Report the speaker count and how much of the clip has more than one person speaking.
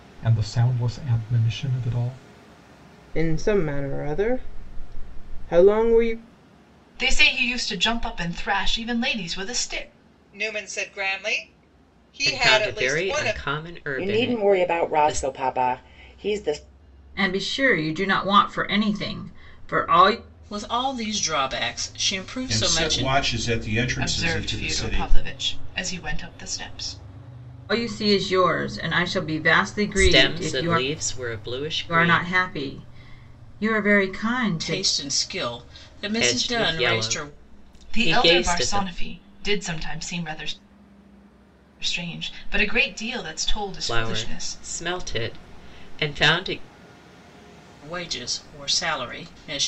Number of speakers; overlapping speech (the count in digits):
9, about 18%